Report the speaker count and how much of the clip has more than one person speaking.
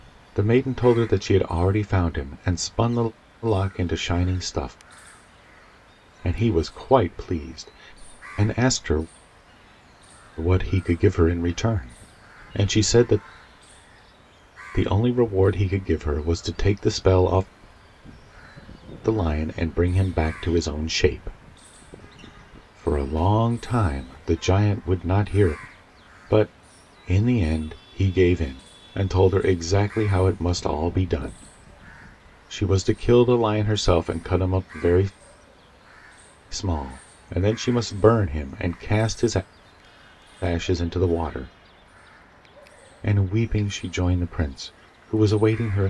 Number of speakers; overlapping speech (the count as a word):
one, no overlap